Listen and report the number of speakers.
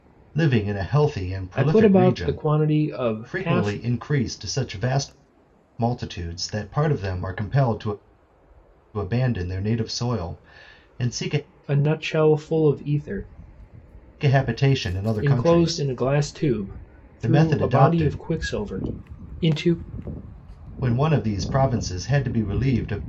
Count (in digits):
2